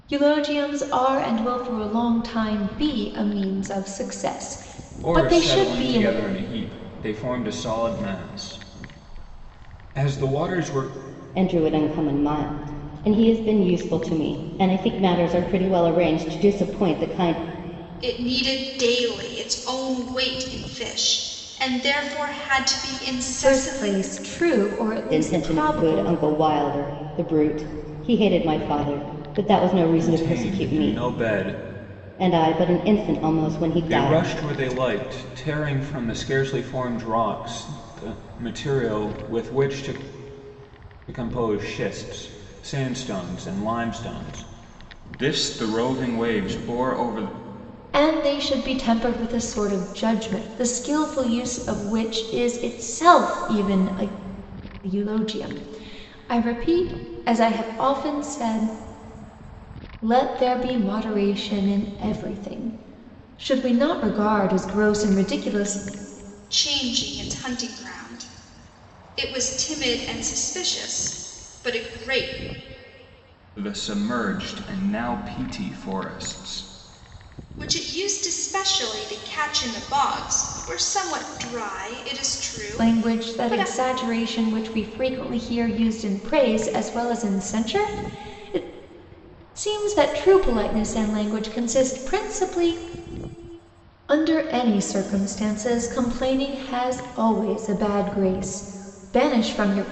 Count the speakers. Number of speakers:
four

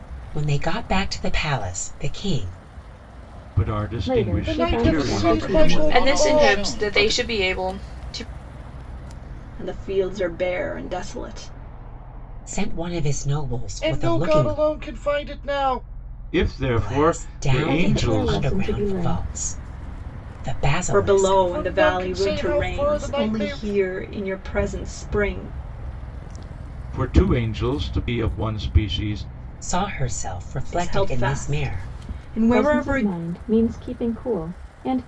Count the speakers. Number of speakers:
eight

